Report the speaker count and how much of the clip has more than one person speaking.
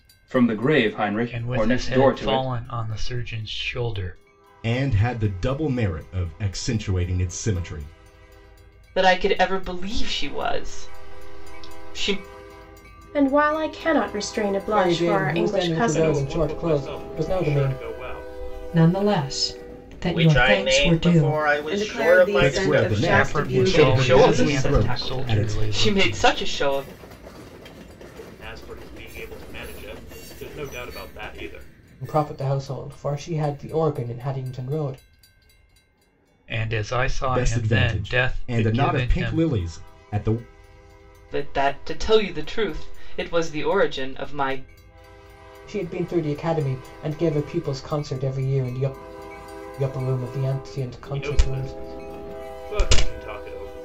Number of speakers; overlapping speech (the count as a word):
ten, about 26%